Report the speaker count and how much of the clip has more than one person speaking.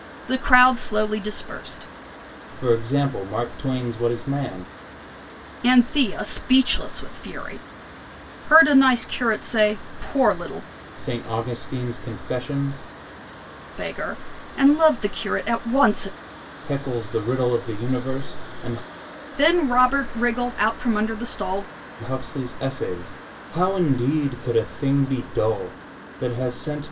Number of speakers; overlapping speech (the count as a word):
two, no overlap